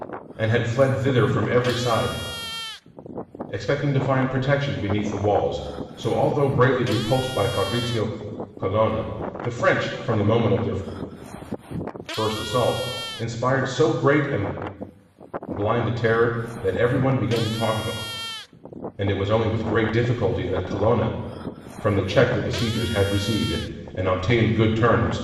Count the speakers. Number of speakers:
1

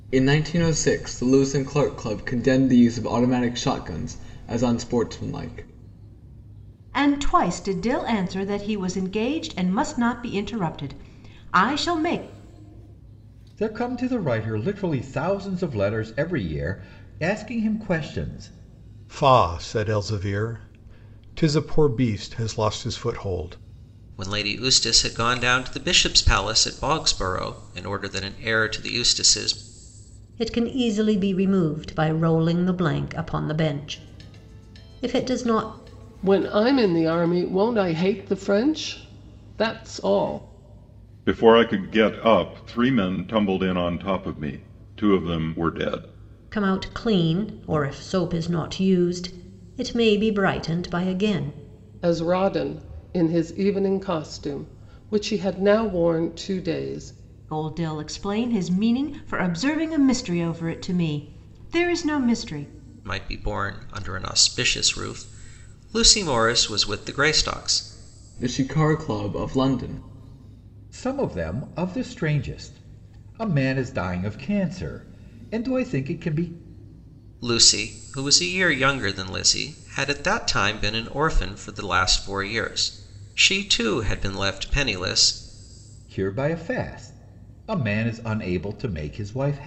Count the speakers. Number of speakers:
8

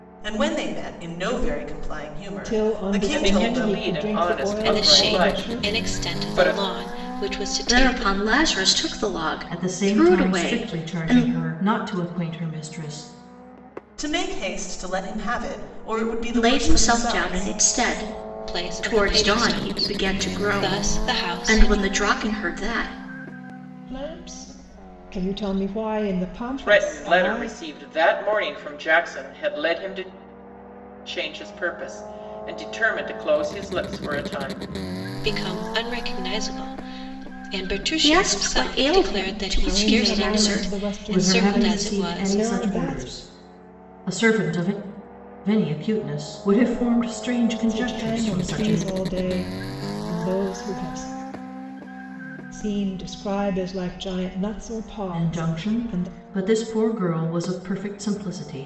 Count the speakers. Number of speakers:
6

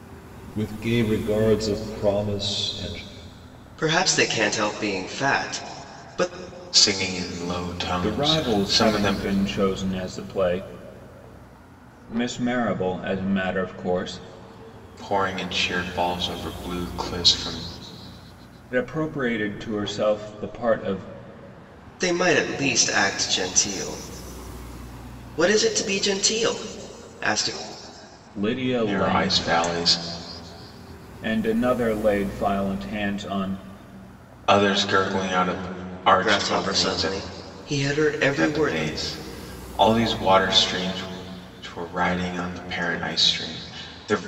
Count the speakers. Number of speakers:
4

